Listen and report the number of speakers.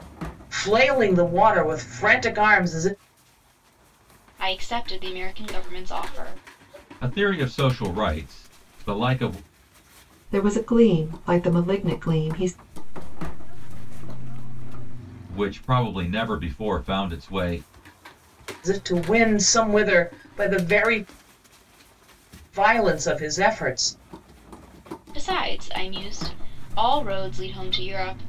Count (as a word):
five